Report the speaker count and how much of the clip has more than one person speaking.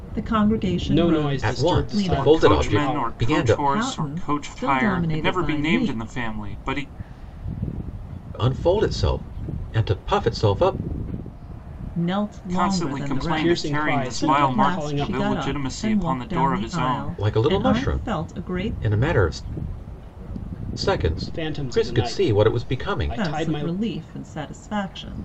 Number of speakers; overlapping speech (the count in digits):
4, about 55%